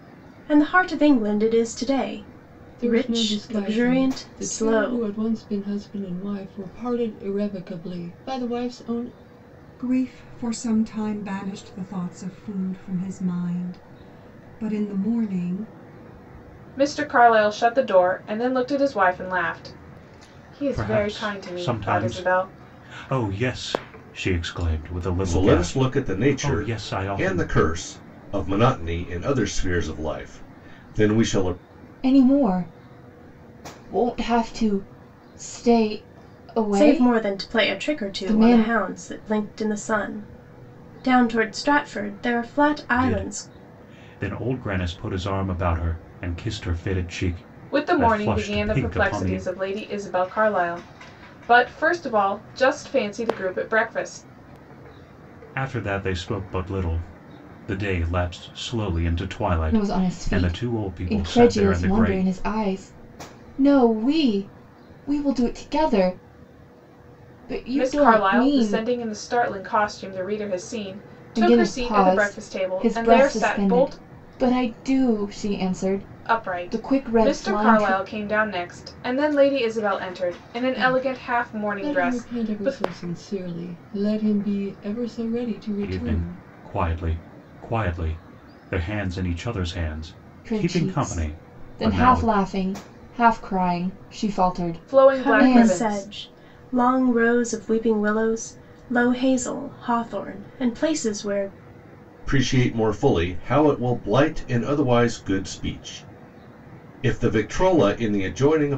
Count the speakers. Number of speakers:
seven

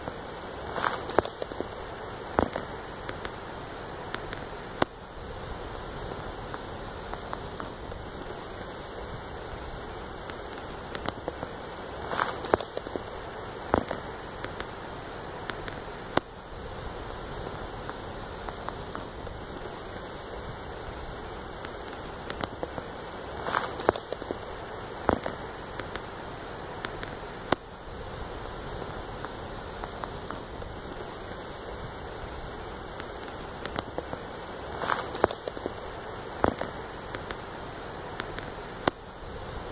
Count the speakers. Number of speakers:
zero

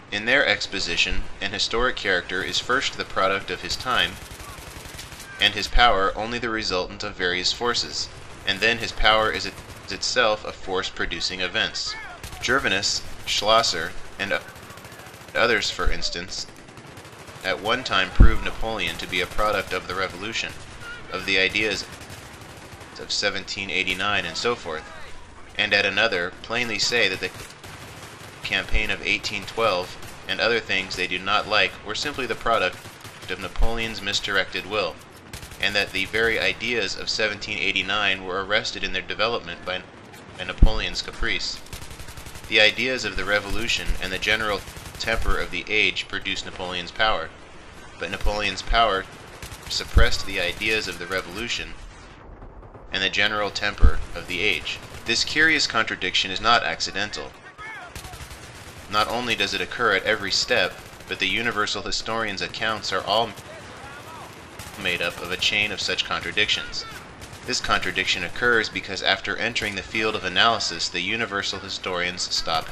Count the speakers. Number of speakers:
one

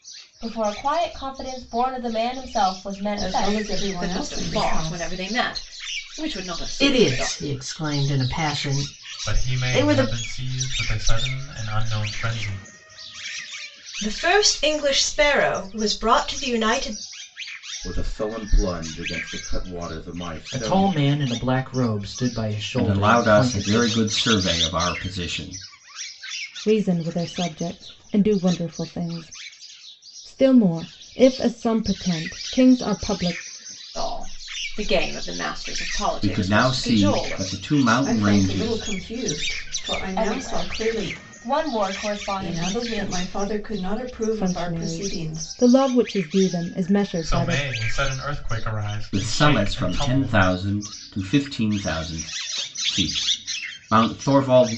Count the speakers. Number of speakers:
ten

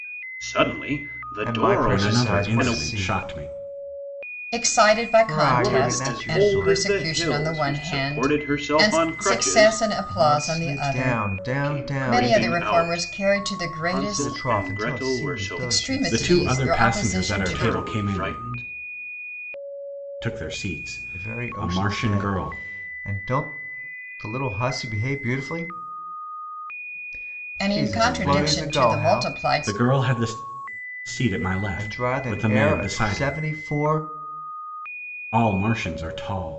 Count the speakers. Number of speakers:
four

